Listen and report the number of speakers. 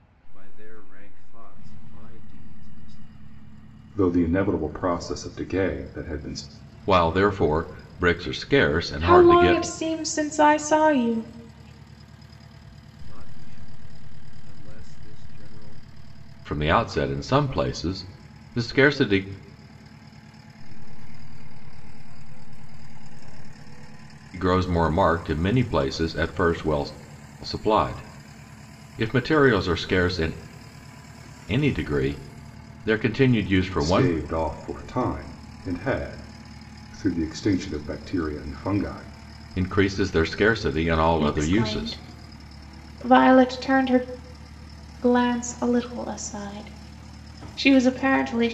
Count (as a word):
four